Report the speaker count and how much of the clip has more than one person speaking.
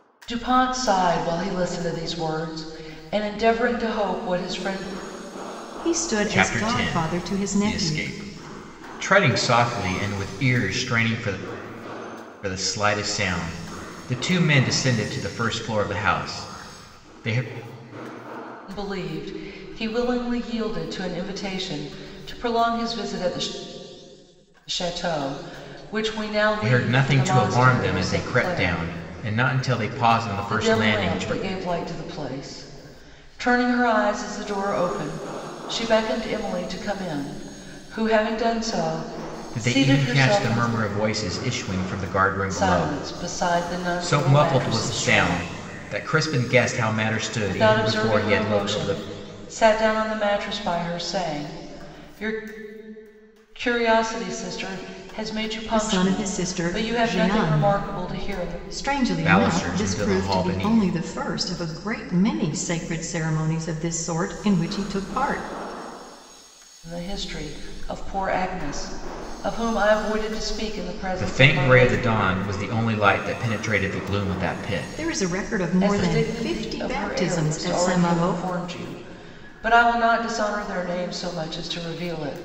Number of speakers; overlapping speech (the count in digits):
3, about 24%